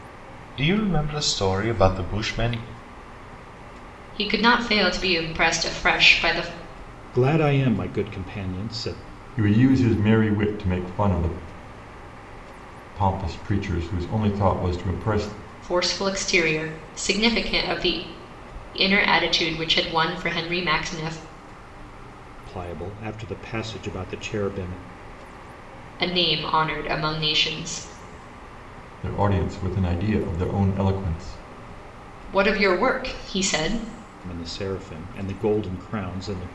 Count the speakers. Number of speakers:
four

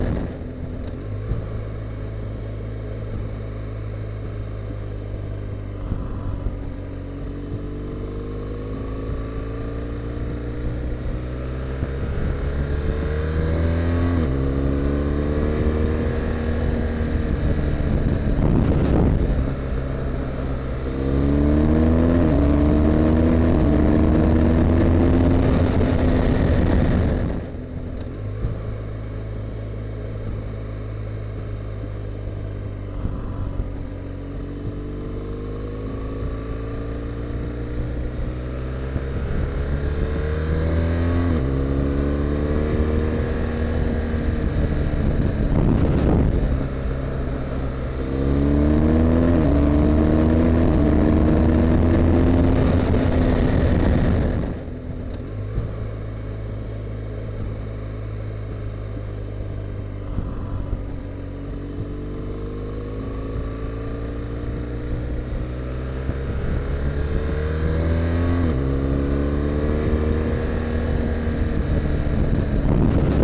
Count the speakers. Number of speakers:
zero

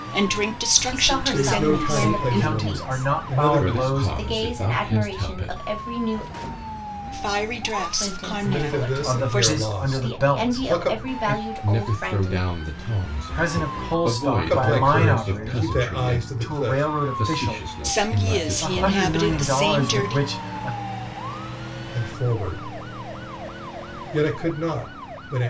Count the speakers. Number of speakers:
five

